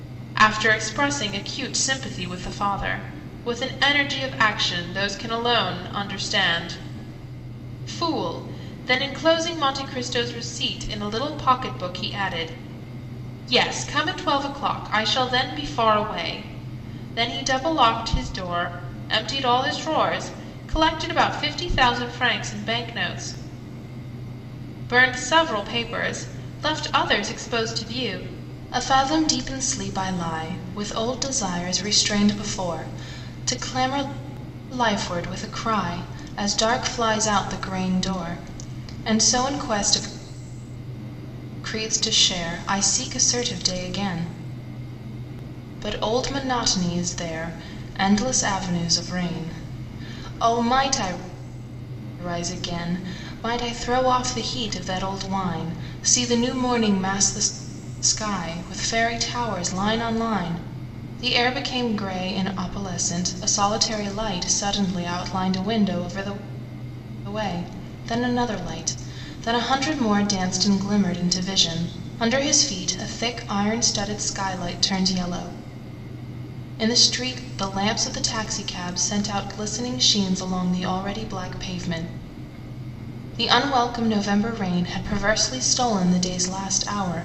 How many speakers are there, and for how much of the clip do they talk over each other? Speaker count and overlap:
1, no overlap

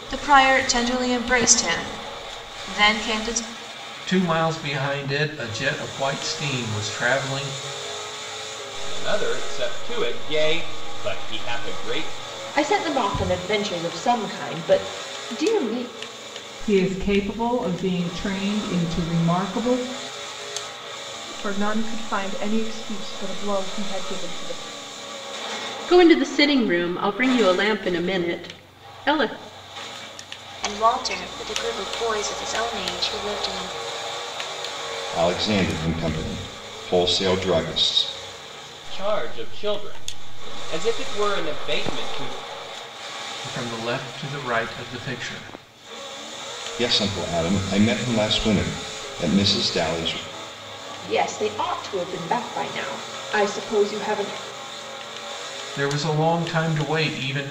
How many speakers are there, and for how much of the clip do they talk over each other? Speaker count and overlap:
9, no overlap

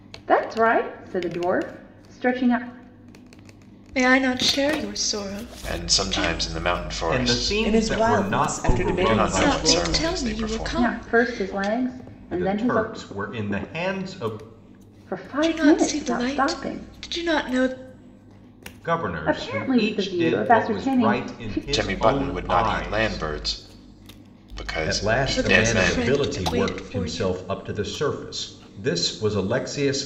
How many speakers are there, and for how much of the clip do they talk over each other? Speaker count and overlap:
5, about 46%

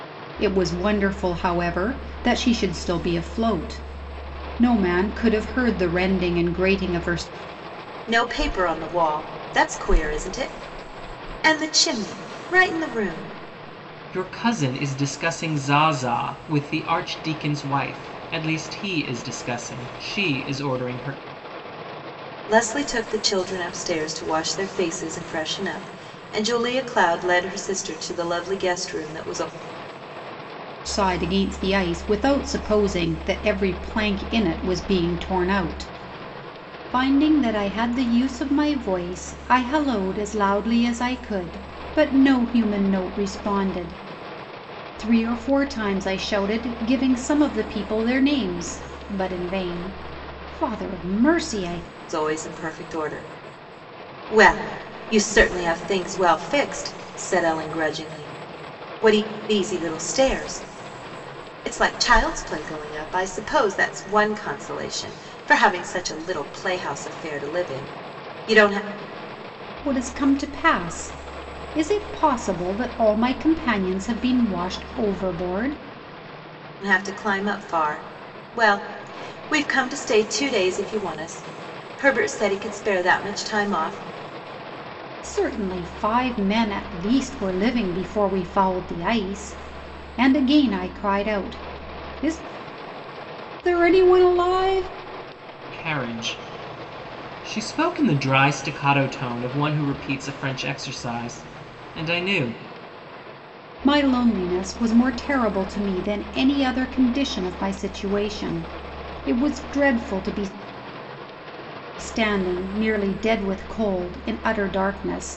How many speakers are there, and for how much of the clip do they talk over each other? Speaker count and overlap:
3, no overlap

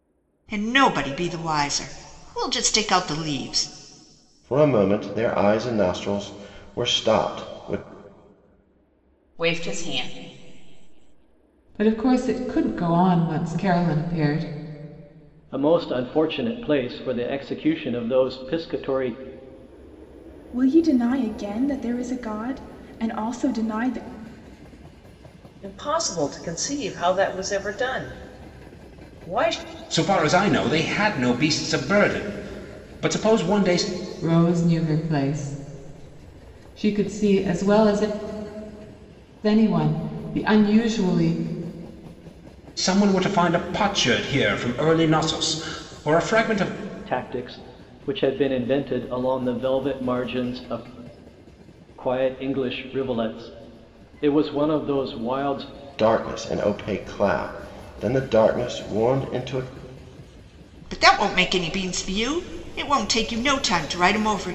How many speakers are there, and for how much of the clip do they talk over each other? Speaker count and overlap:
8, no overlap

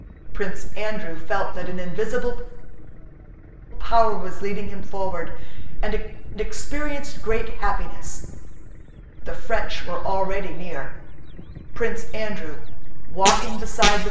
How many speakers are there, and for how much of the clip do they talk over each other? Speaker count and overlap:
1, no overlap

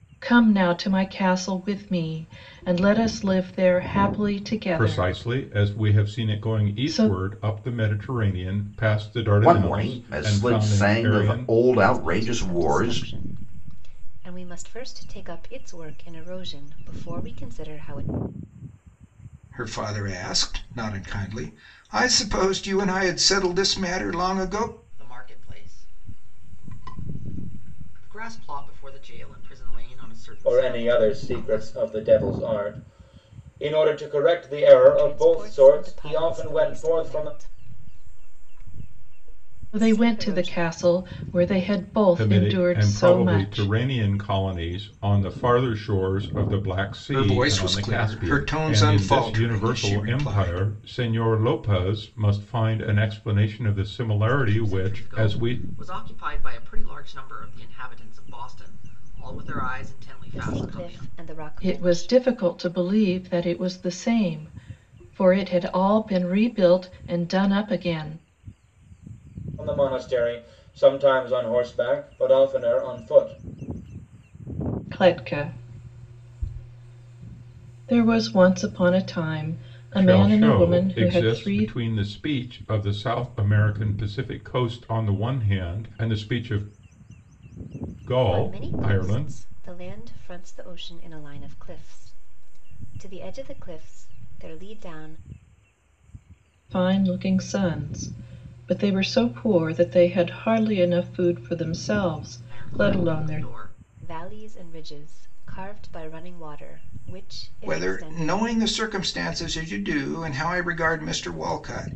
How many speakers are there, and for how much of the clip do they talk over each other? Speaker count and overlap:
7, about 20%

